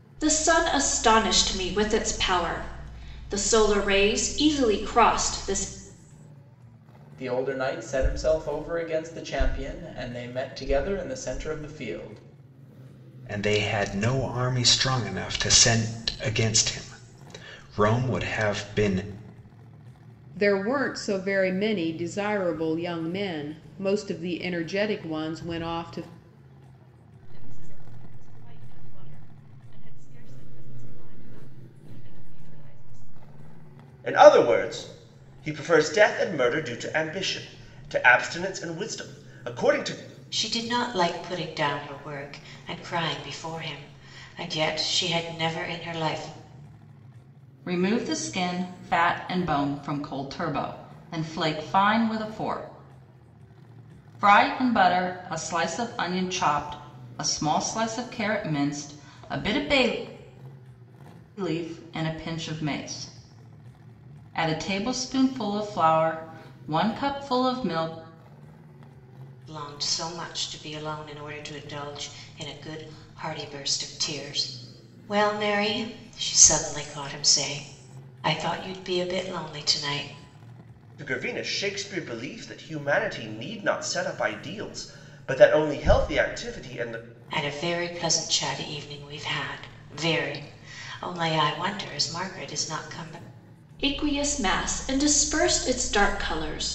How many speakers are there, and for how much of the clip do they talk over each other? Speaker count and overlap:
8, no overlap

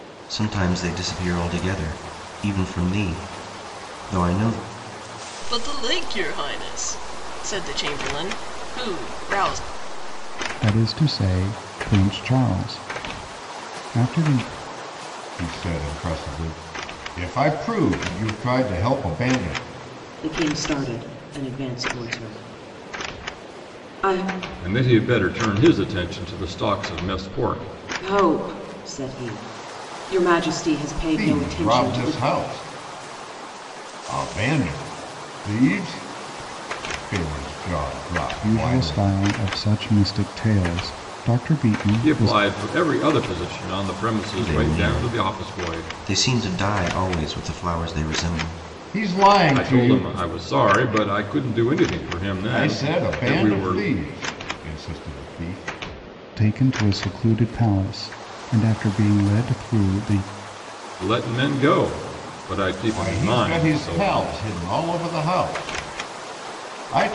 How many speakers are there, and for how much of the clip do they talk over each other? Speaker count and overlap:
6, about 11%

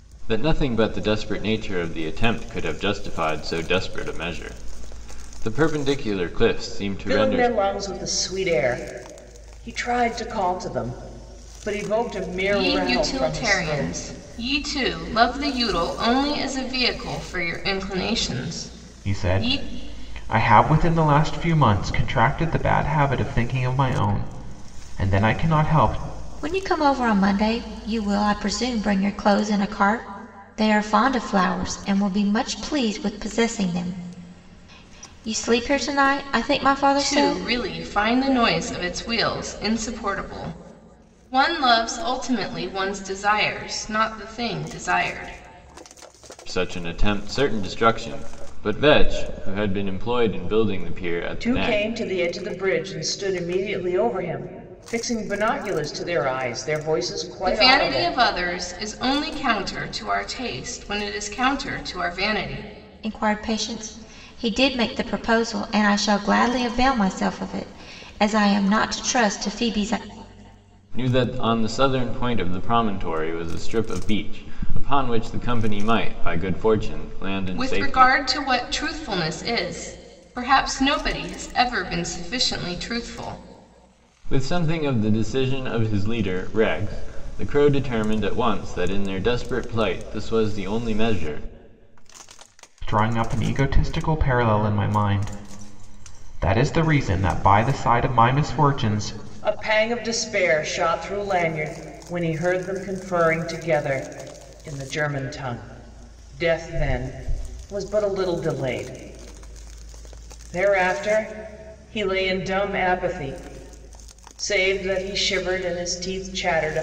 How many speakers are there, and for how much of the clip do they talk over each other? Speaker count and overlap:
5, about 4%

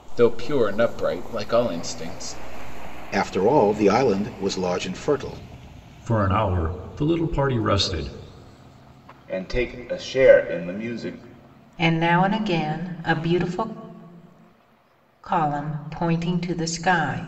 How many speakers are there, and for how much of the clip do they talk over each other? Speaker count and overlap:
5, no overlap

